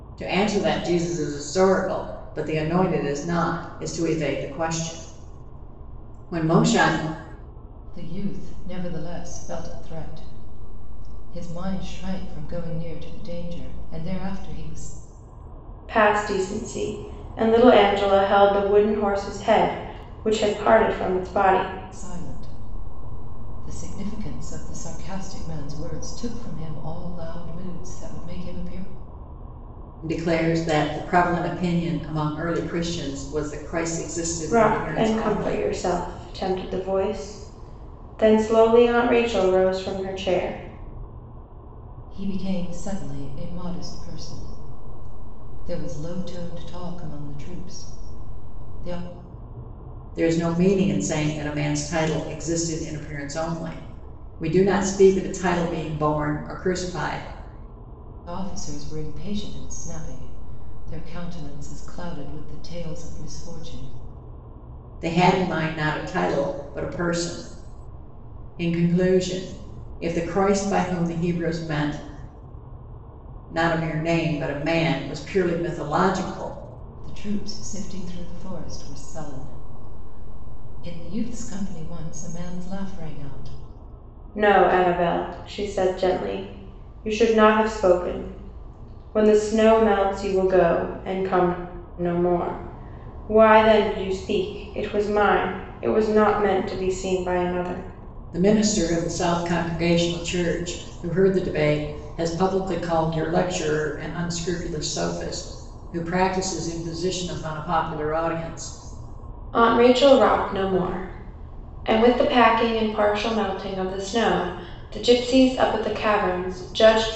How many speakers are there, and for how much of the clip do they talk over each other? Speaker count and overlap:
three, about 1%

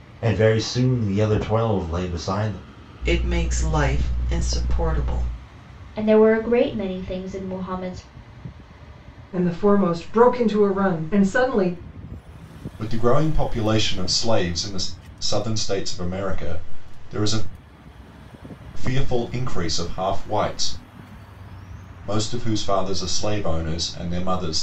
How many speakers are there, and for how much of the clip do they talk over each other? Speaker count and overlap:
five, no overlap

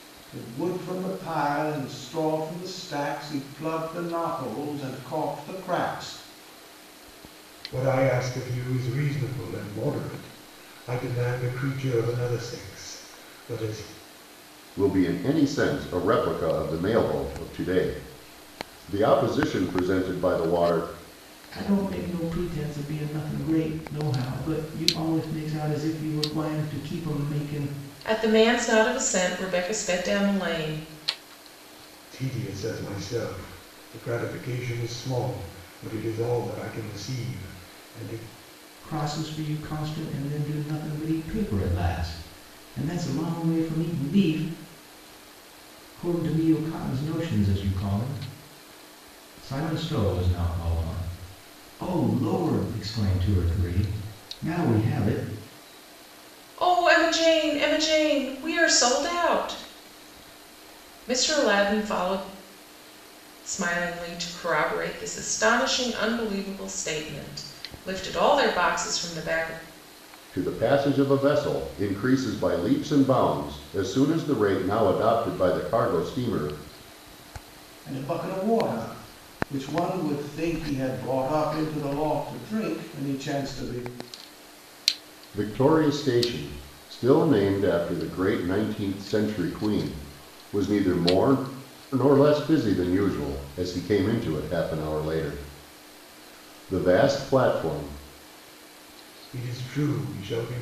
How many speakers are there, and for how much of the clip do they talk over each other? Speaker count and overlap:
five, no overlap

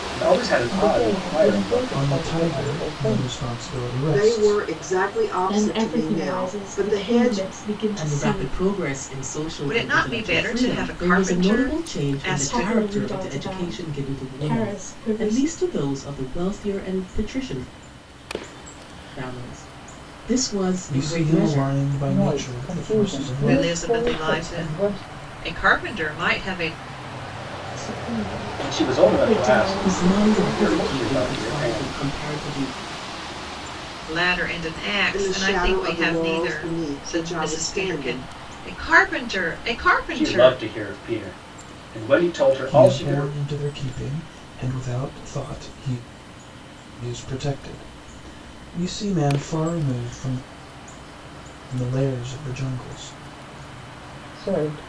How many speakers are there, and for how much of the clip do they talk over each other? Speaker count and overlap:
seven, about 44%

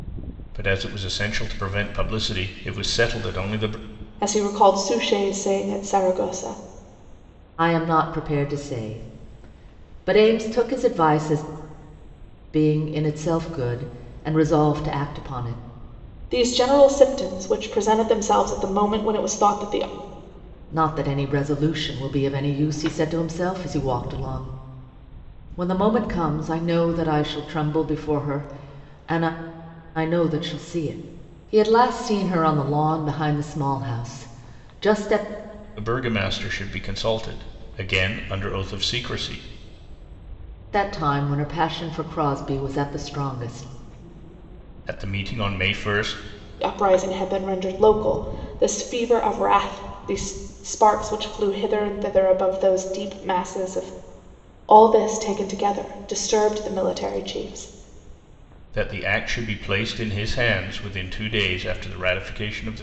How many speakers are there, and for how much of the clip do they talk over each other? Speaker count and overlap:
three, no overlap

